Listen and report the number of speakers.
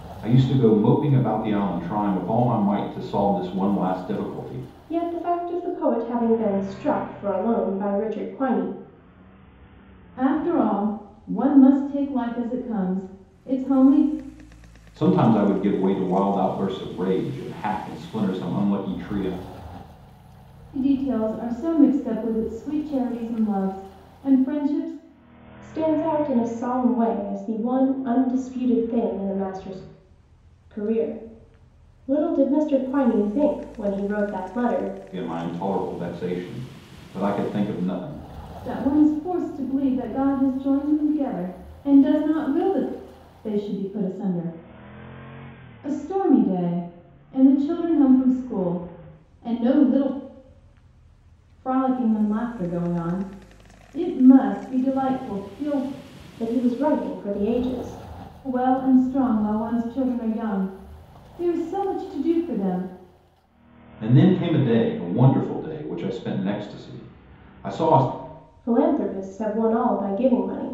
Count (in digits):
3